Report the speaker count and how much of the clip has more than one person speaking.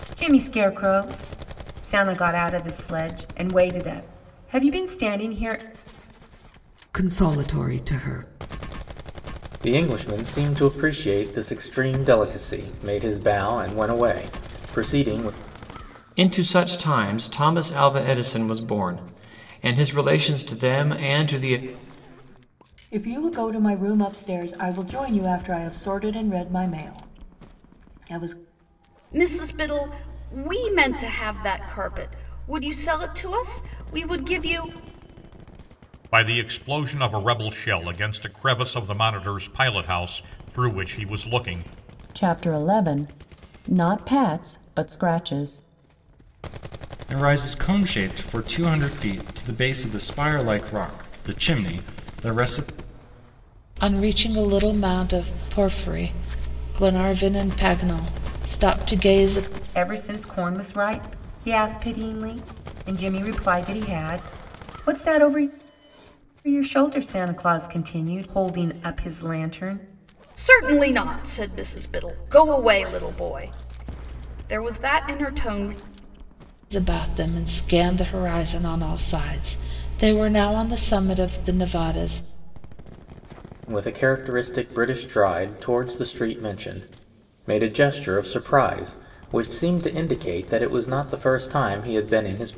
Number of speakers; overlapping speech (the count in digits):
10, no overlap